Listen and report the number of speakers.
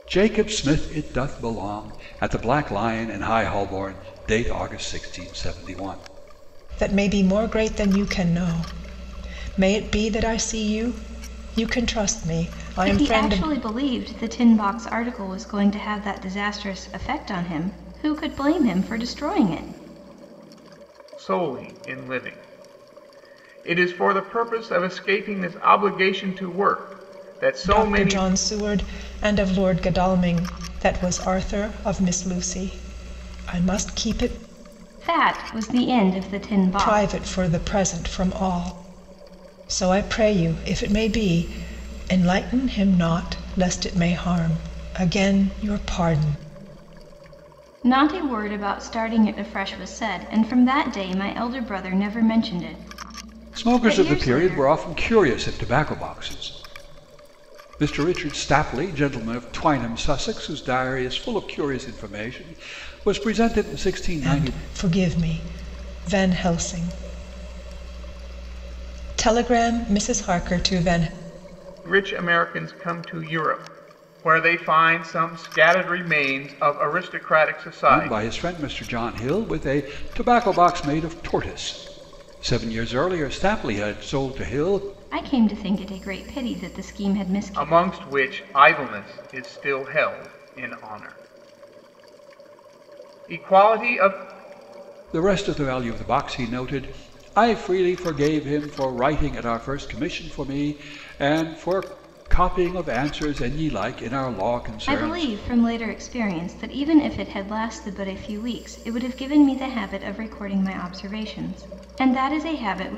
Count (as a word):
four